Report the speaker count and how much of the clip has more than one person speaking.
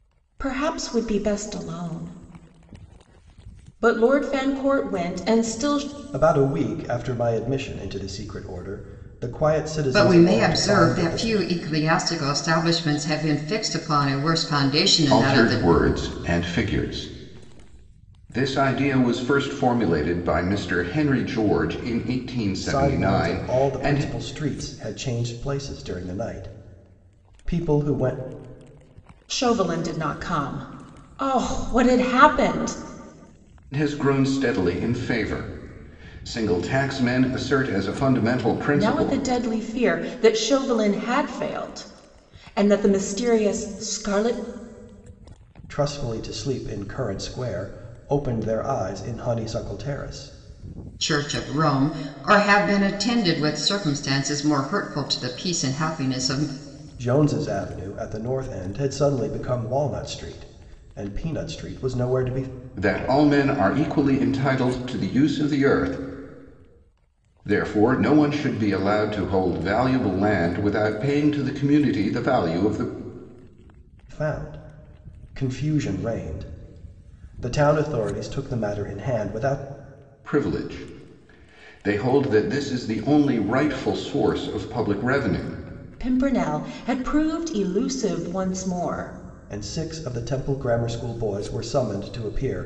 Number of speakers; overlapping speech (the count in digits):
4, about 4%